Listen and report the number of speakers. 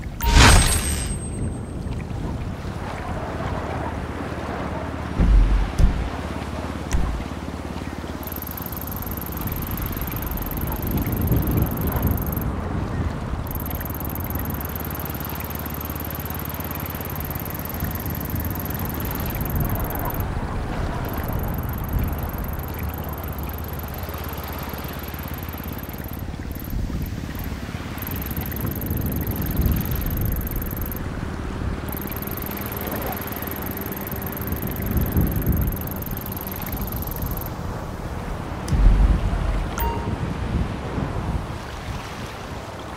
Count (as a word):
zero